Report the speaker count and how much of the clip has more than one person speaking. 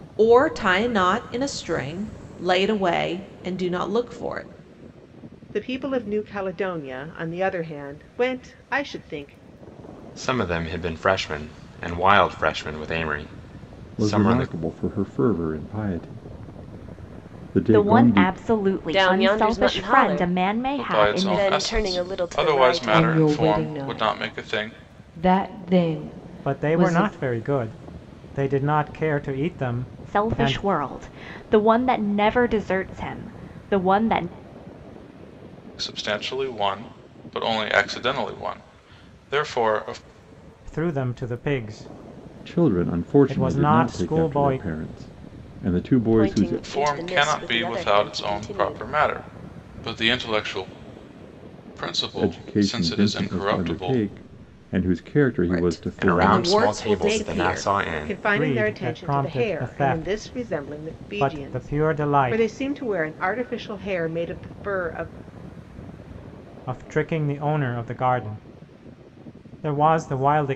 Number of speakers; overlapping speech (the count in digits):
9, about 32%